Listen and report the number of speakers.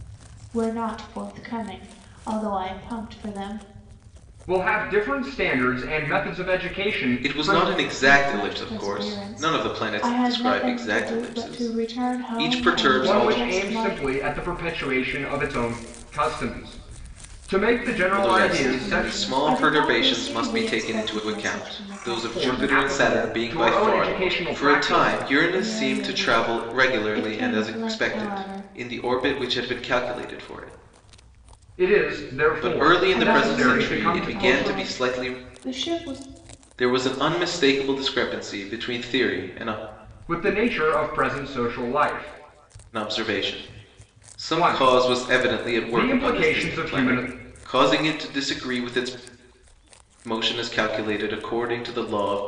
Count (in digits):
3